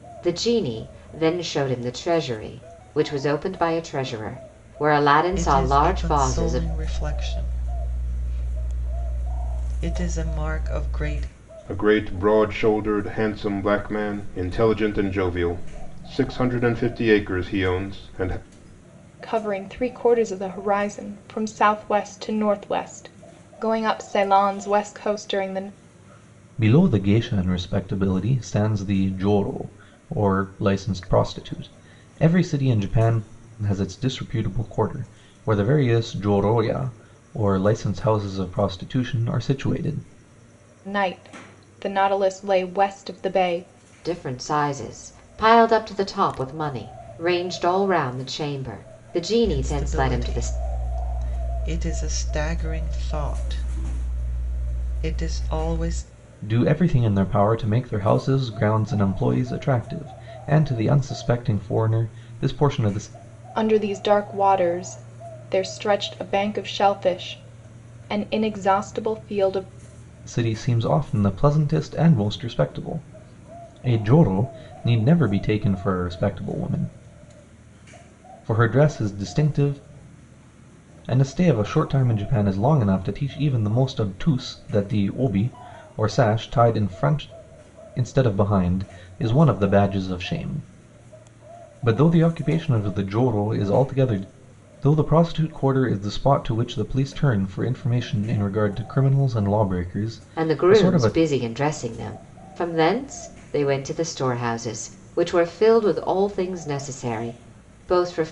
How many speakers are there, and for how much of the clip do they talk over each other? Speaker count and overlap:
5, about 3%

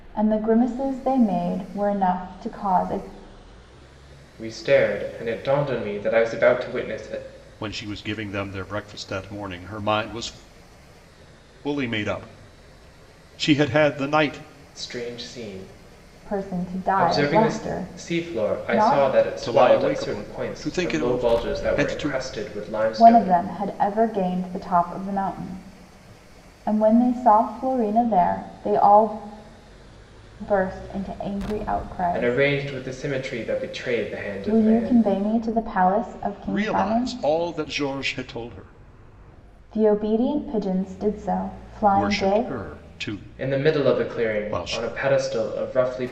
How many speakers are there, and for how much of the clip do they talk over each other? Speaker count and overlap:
3, about 20%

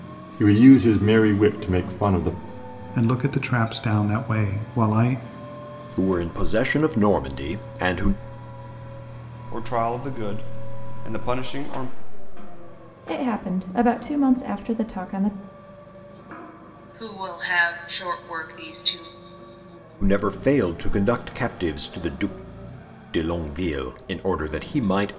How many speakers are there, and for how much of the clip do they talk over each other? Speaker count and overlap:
6, no overlap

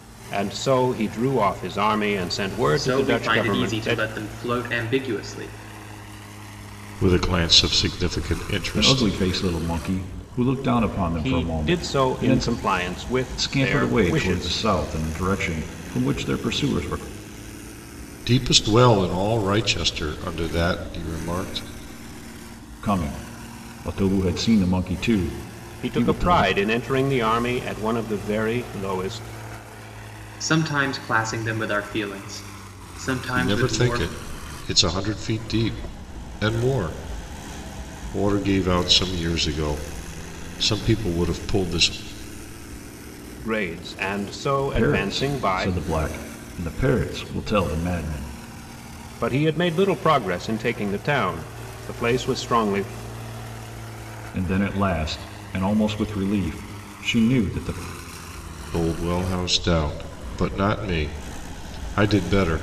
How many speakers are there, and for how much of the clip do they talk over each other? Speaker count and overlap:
4, about 11%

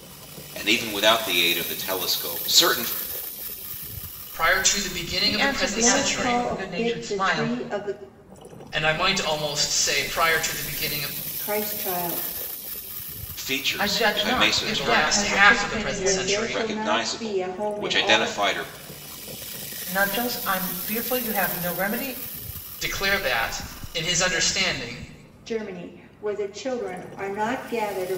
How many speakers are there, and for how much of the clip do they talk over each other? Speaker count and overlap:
4, about 24%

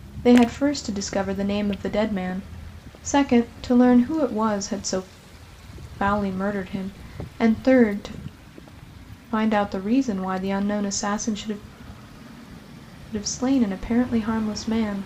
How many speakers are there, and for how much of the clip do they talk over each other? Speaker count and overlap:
1, no overlap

